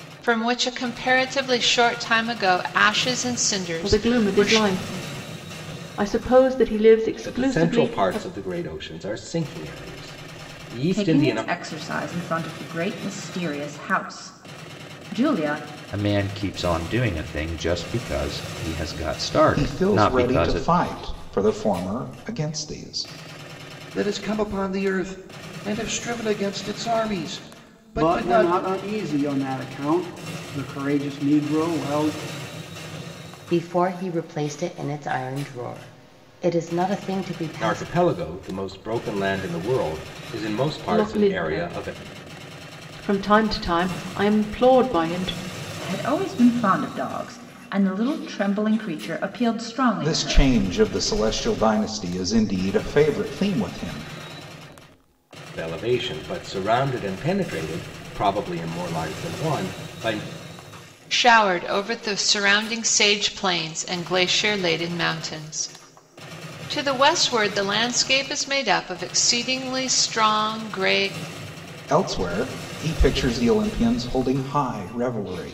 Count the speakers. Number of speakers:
9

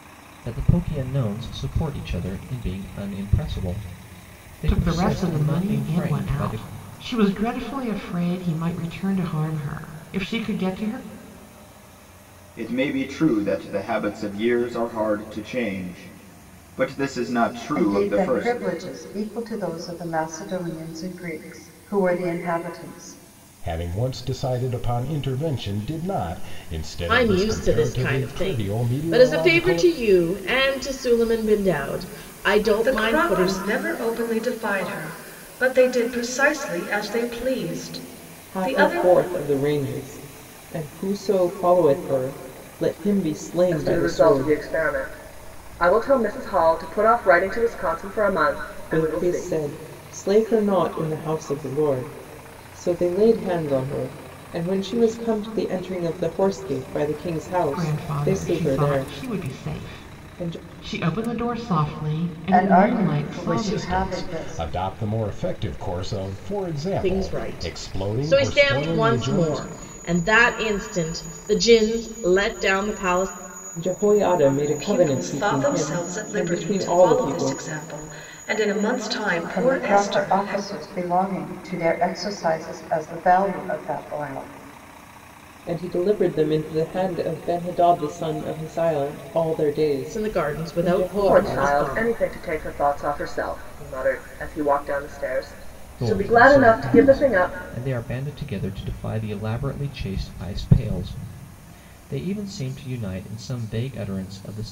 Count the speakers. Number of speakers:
9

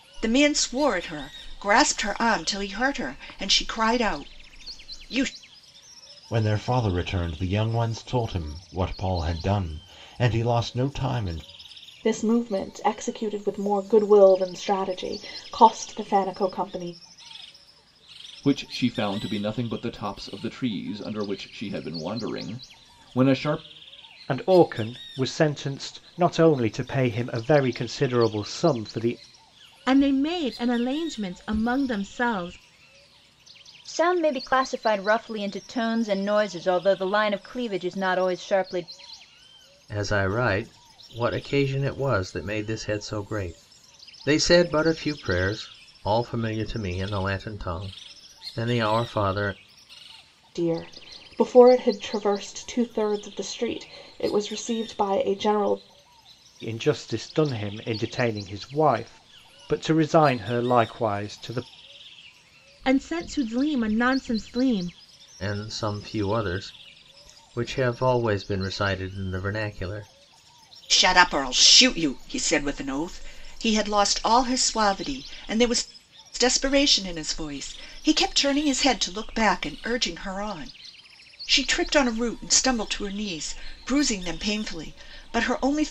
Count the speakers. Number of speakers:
8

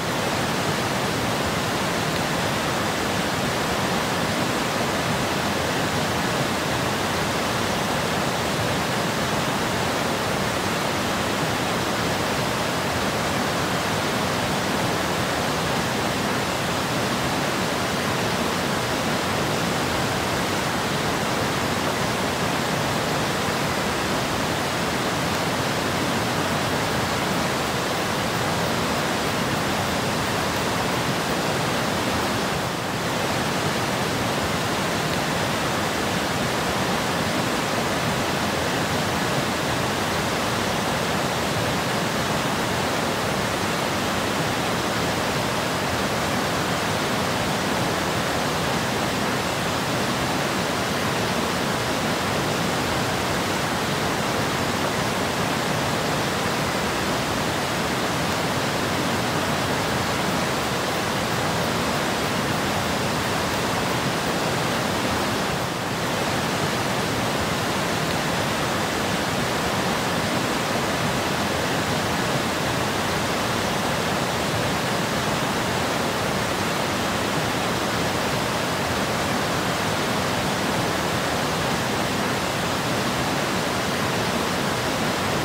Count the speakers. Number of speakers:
0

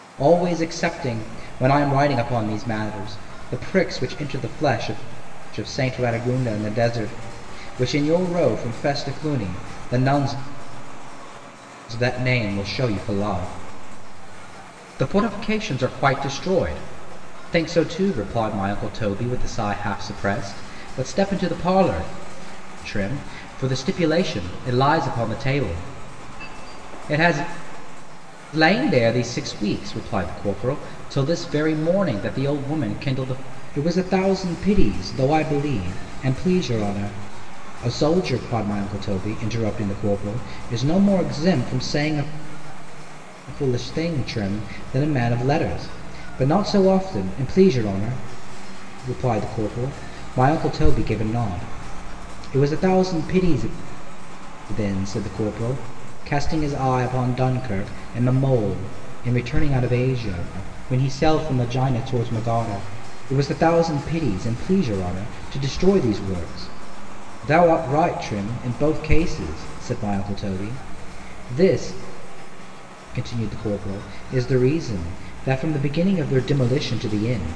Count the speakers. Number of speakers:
1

